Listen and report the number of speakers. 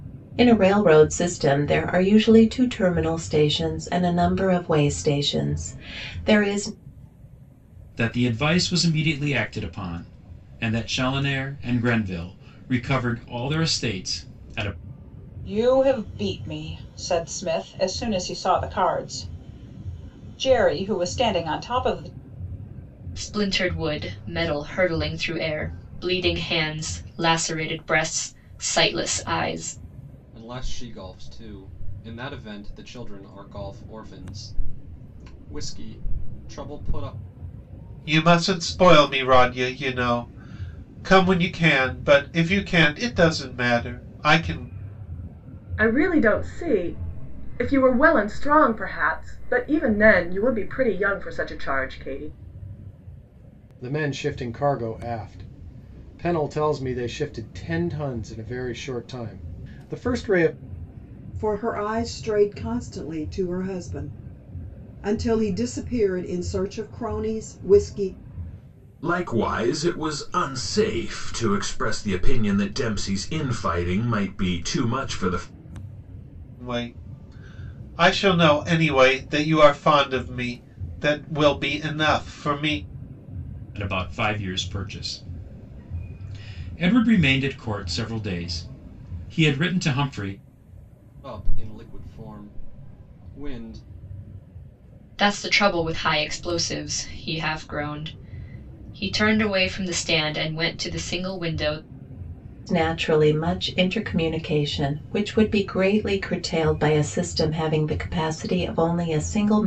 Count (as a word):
ten